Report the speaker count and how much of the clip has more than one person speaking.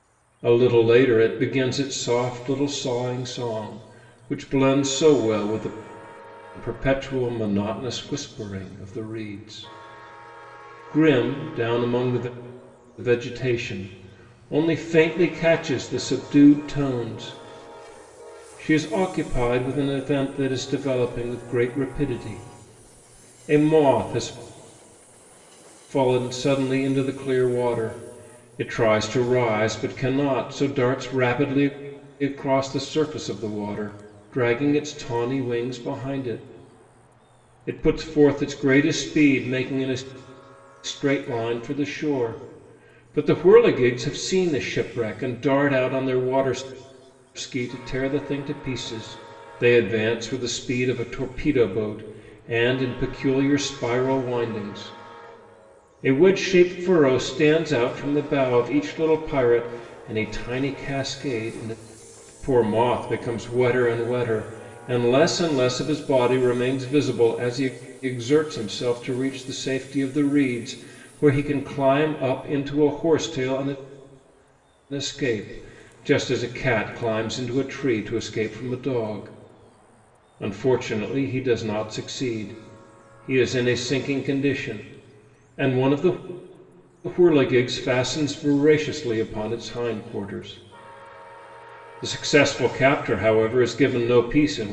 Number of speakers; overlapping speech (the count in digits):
1, no overlap